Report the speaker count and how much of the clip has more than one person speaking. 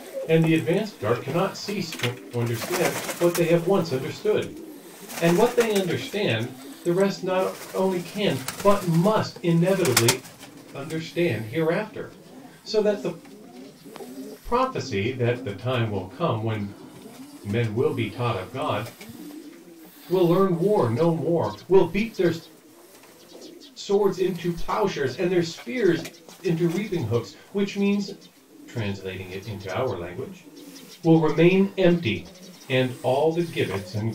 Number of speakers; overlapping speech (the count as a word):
one, no overlap